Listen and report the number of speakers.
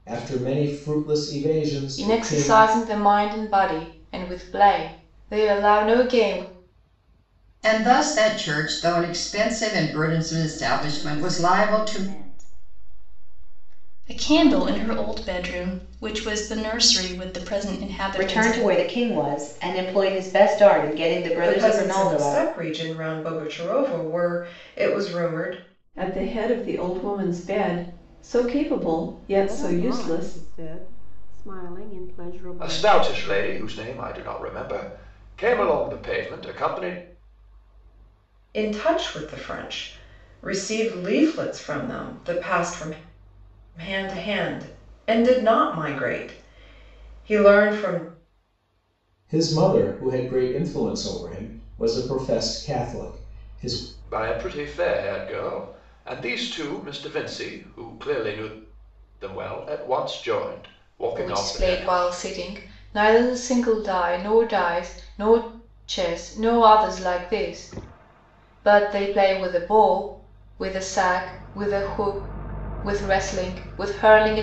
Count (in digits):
10